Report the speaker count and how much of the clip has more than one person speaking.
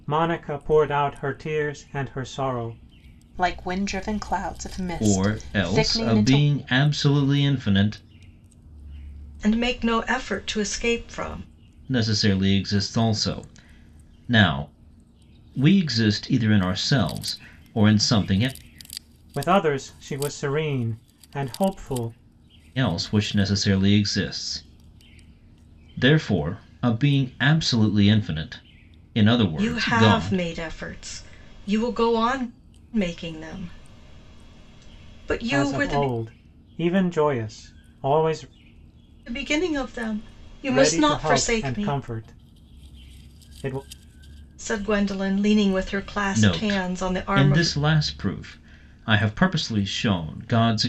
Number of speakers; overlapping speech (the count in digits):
4, about 11%